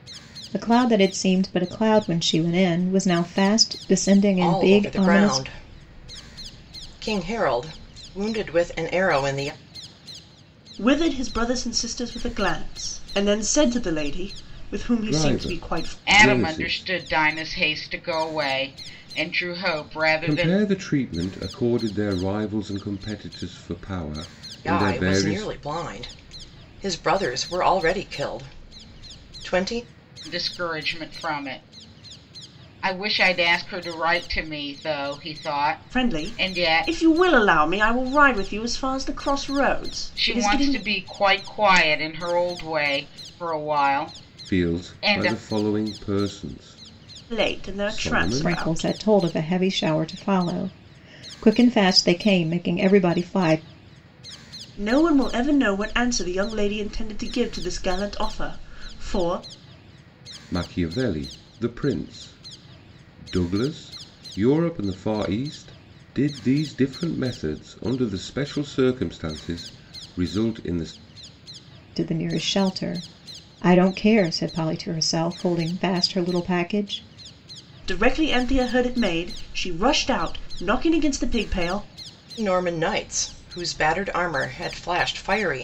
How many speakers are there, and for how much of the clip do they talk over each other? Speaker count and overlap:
5, about 10%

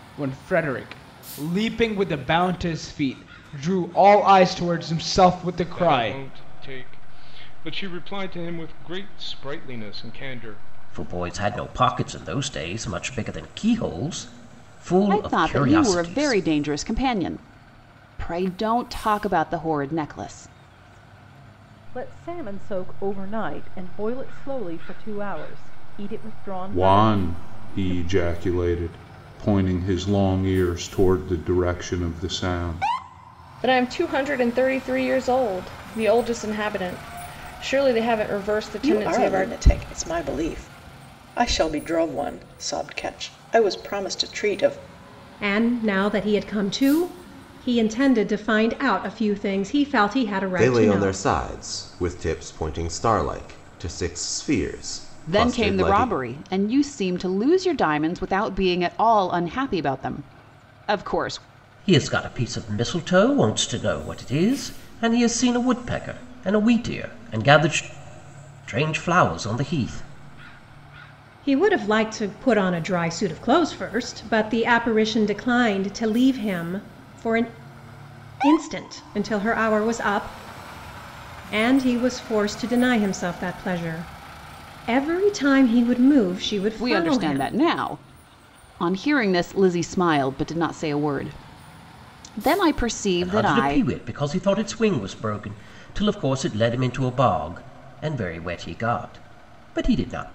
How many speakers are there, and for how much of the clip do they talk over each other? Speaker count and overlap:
10, about 7%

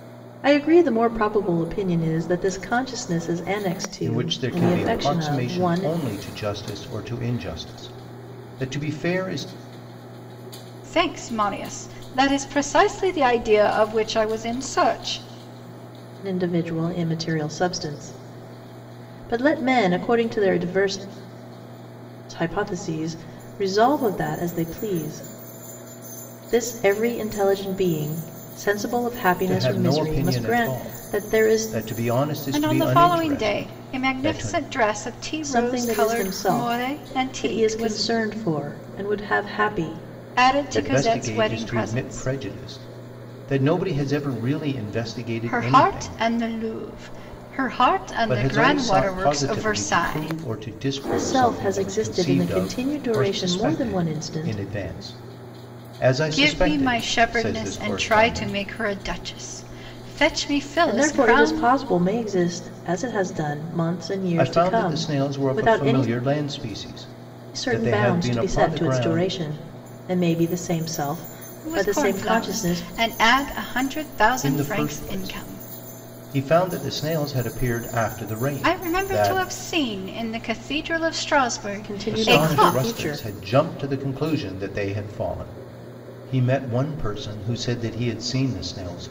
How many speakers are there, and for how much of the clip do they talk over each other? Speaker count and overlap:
3, about 33%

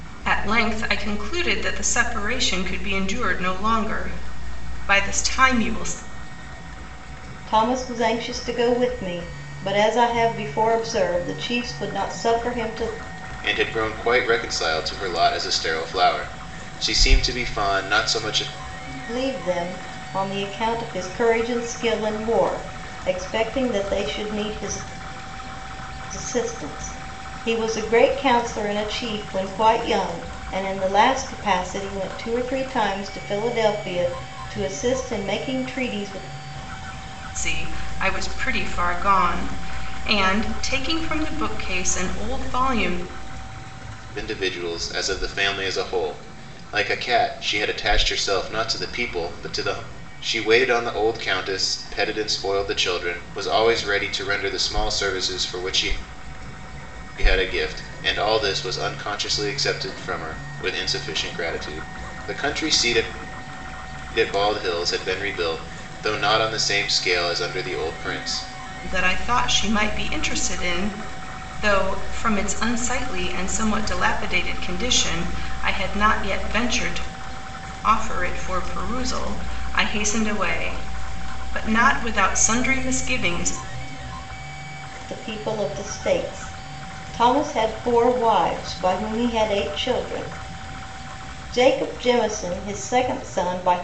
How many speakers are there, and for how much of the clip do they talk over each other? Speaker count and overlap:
3, no overlap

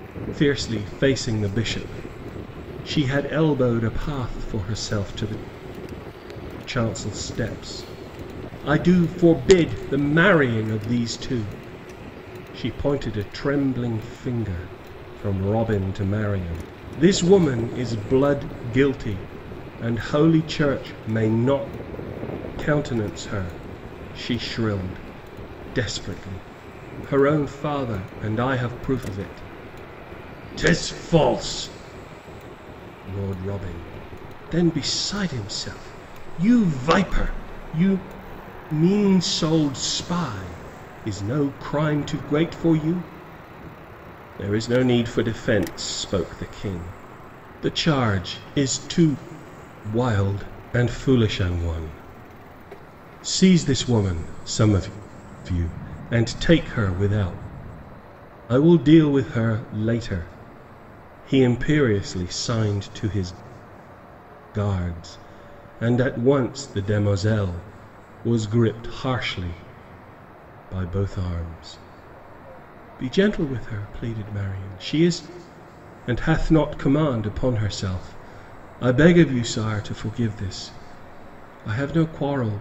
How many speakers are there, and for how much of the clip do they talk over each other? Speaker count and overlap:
1, no overlap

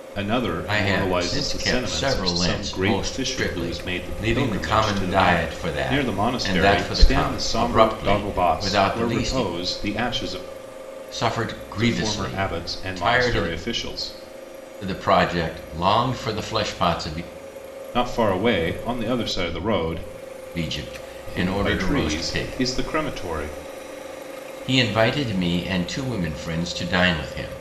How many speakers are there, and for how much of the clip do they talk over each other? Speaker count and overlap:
2, about 42%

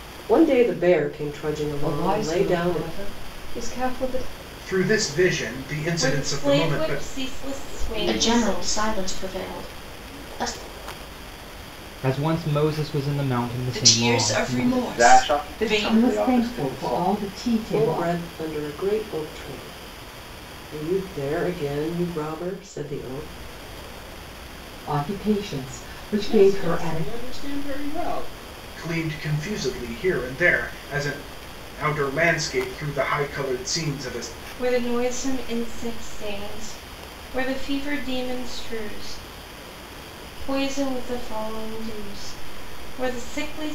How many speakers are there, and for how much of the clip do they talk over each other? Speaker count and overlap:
10, about 20%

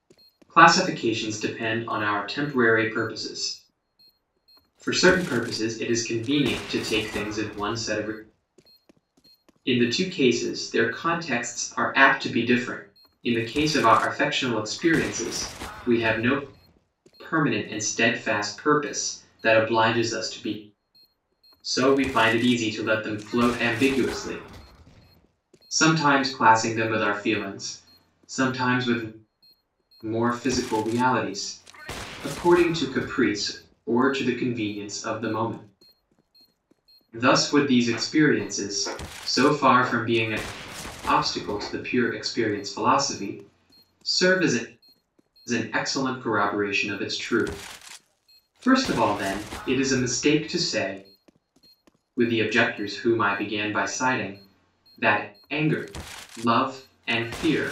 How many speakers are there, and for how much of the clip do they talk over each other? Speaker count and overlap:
1, no overlap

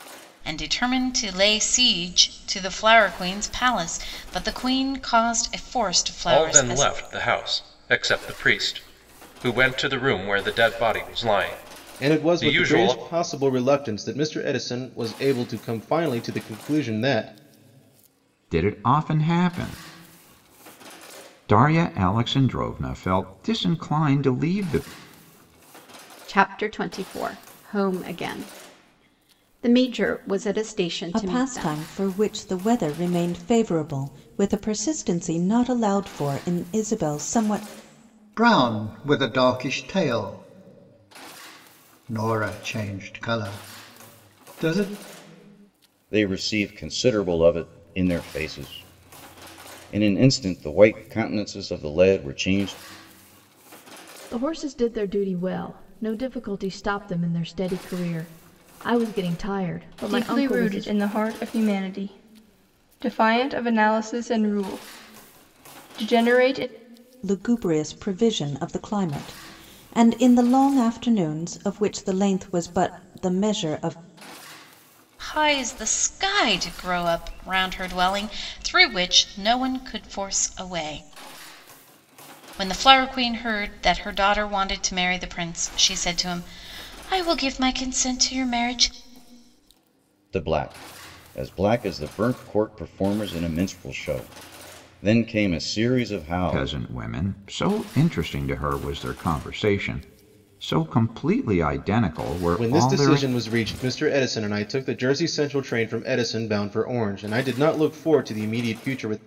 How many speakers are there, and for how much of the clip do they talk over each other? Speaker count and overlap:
10, about 4%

